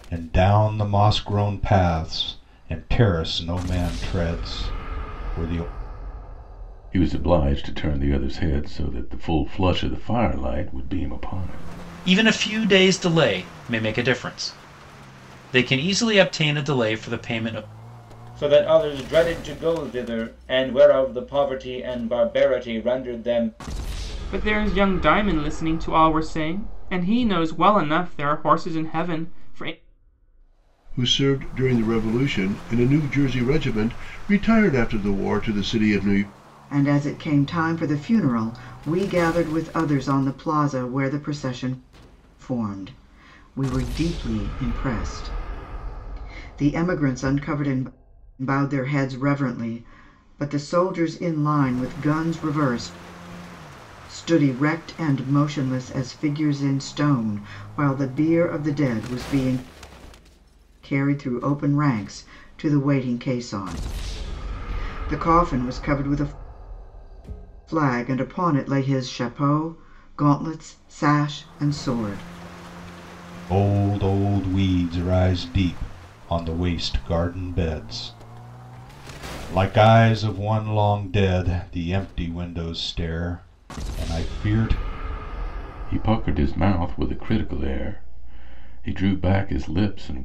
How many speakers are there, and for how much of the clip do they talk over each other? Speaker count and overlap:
seven, no overlap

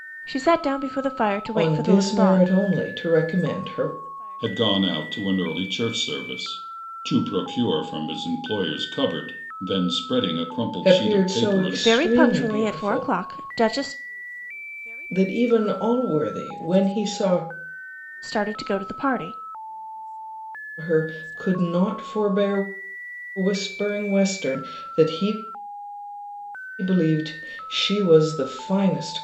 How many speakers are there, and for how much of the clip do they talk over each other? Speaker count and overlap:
three, about 11%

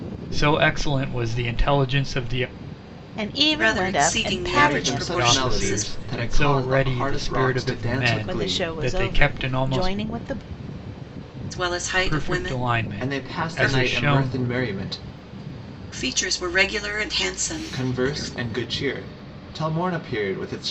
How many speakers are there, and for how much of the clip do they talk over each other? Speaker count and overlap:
four, about 46%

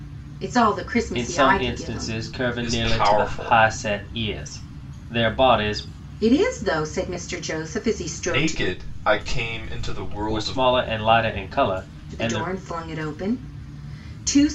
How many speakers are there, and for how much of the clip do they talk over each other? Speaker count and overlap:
three, about 23%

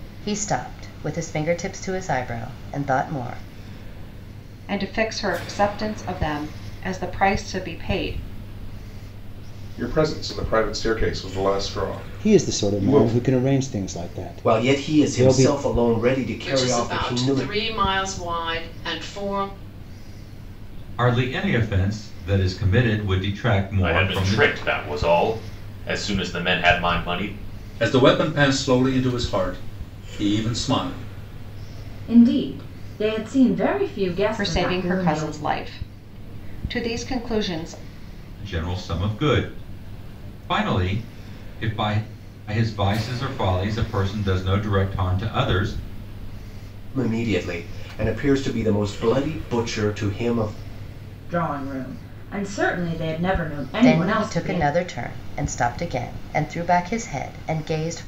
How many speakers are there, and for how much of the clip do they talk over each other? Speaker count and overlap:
ten, about 10%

